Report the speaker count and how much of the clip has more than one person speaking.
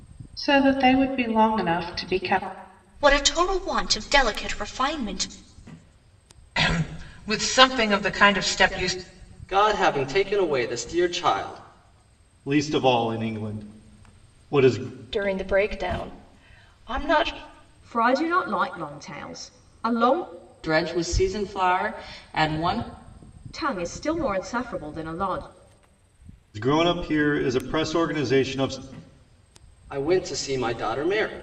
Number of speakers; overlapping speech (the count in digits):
8, no overlap